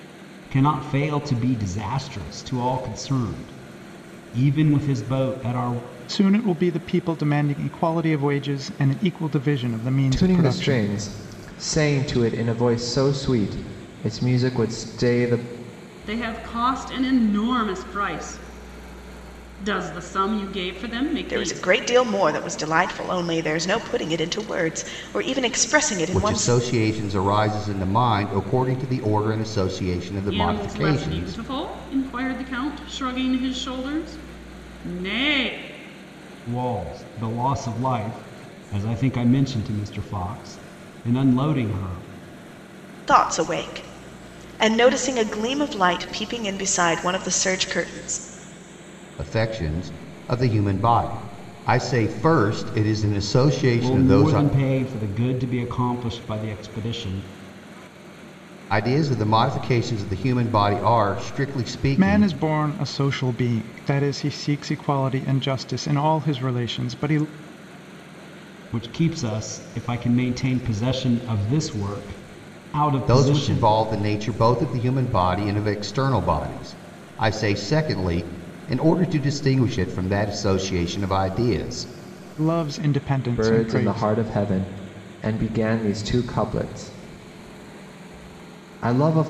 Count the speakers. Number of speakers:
six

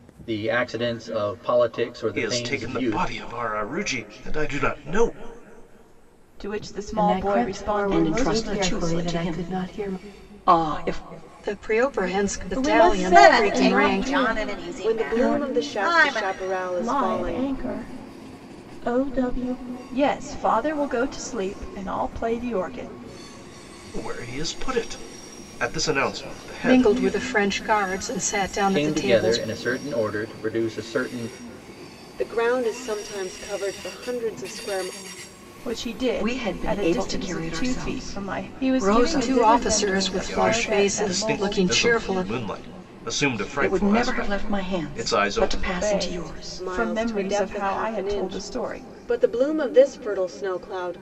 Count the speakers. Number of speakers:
nine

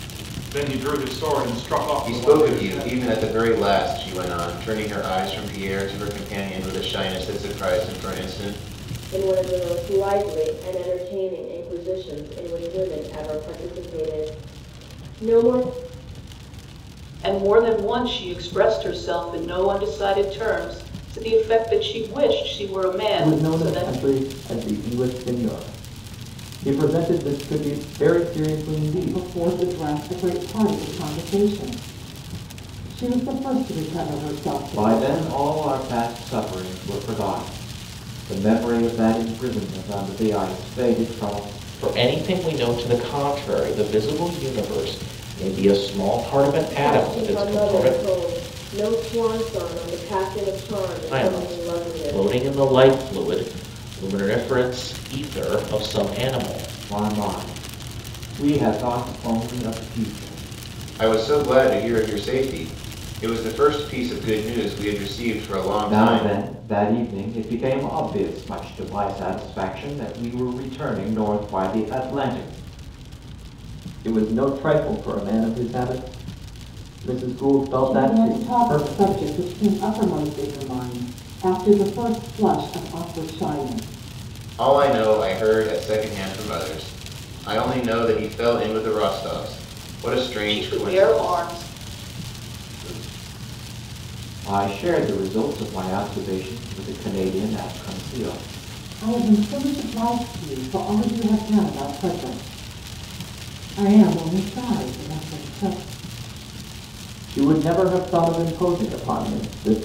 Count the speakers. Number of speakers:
eight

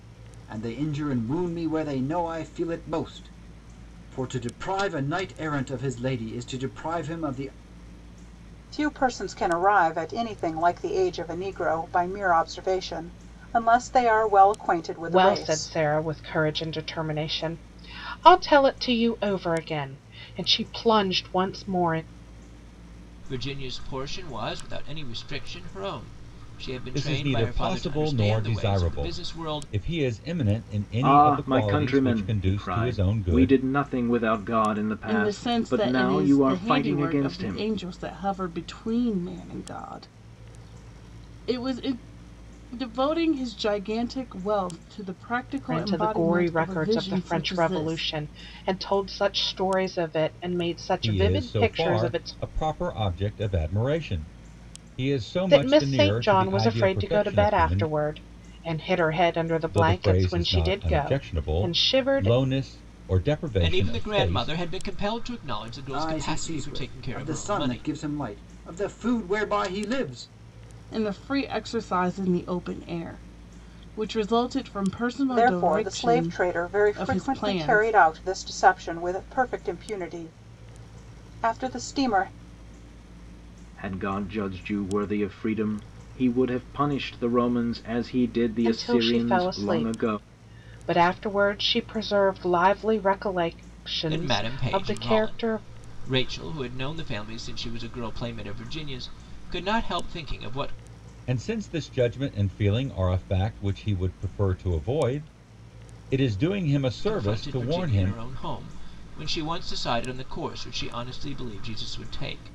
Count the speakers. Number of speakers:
seven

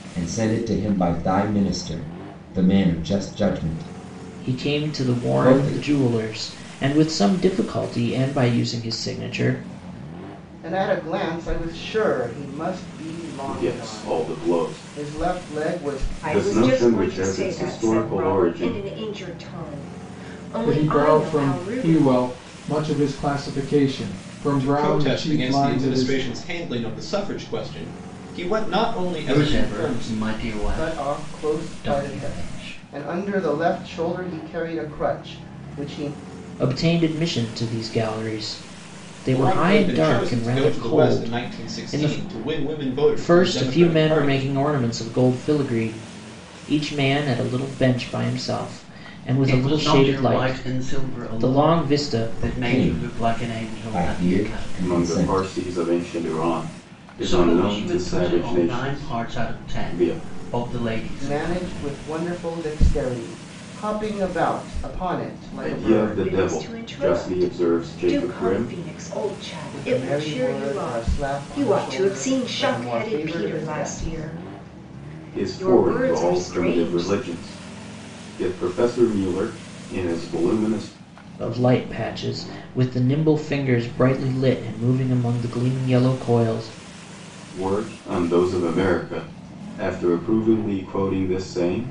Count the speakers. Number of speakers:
eight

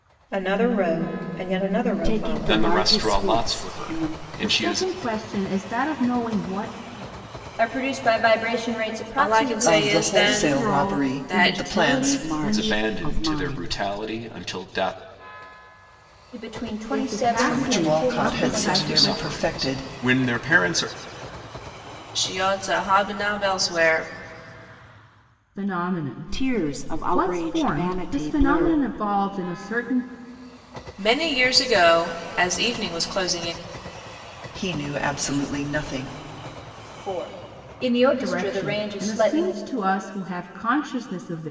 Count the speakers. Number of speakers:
seven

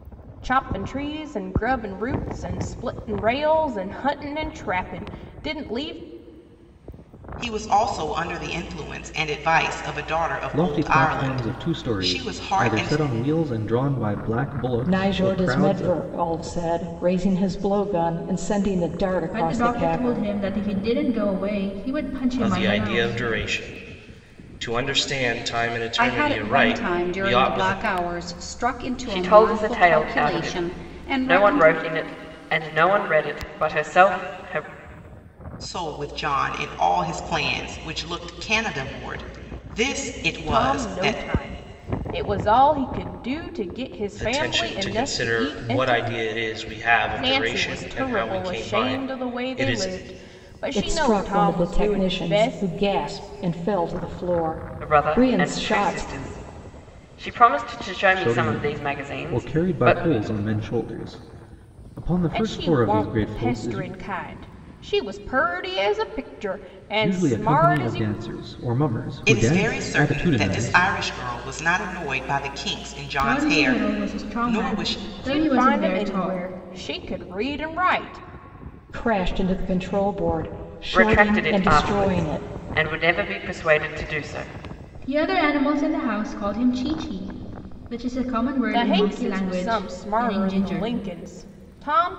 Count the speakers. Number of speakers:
eight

